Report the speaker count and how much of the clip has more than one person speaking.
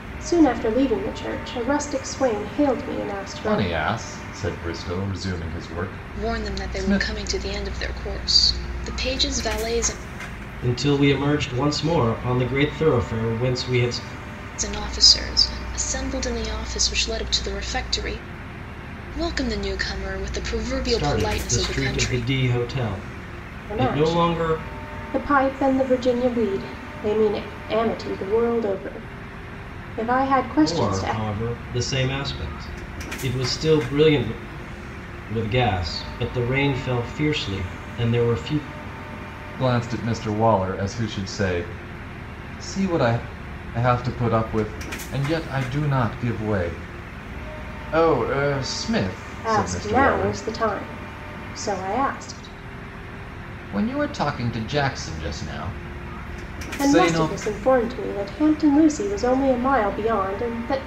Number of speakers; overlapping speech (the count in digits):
4, about 9%